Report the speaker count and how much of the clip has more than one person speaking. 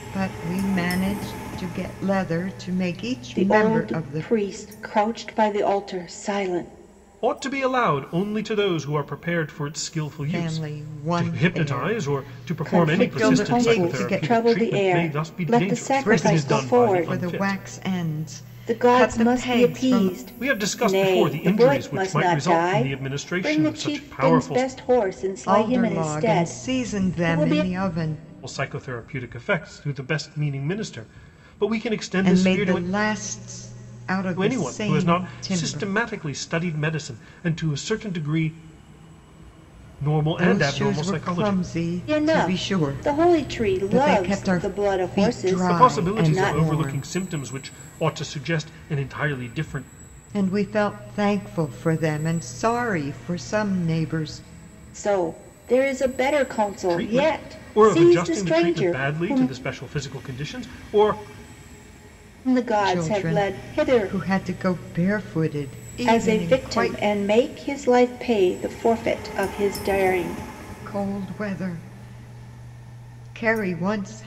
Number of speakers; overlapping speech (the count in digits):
3, about 39%